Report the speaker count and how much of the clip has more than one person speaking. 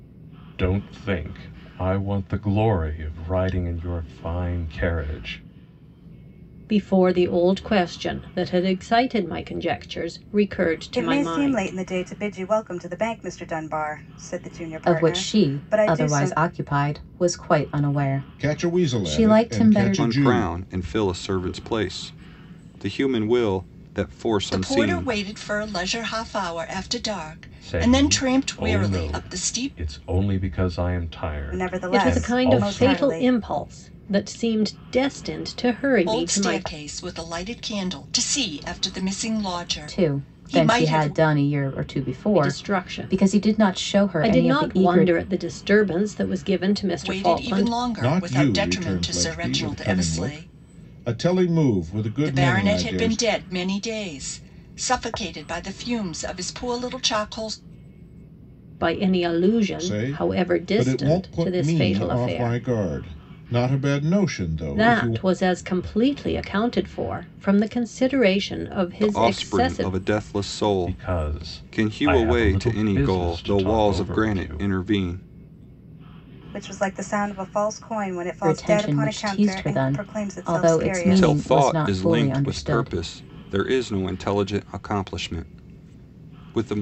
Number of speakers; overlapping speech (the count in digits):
7, about 36%